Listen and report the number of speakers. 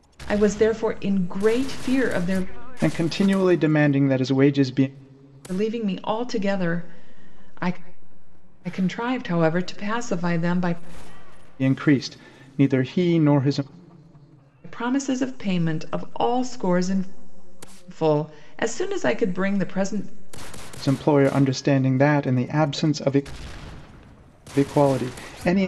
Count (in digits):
2